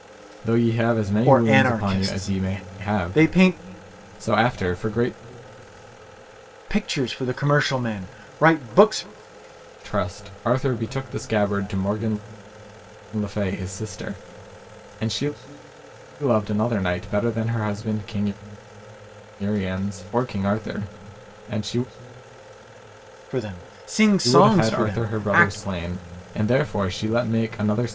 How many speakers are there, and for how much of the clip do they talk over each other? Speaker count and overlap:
2, about 13%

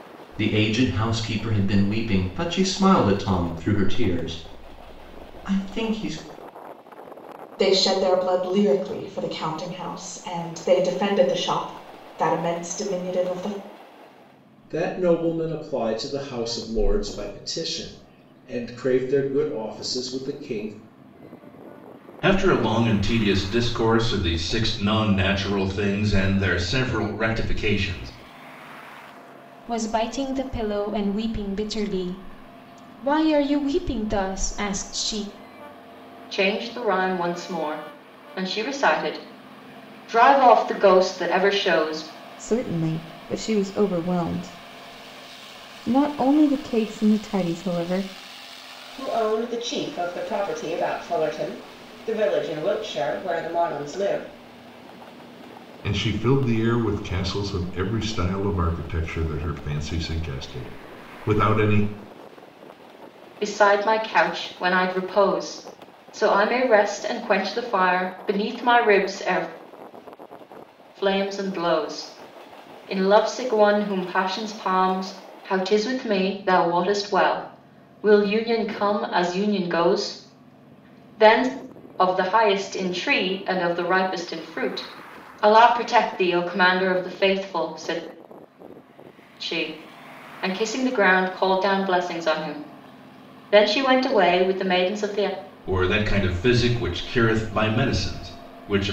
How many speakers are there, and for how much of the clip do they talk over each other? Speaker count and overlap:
9, no overlap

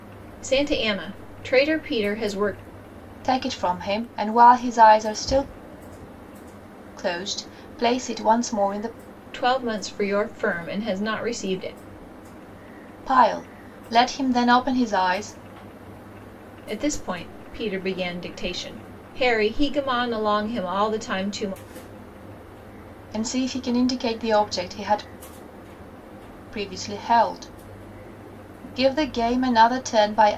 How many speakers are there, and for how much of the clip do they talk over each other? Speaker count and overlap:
2, no overlap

